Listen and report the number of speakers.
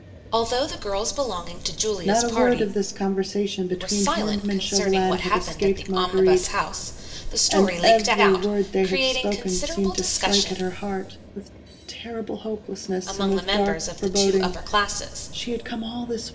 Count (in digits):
2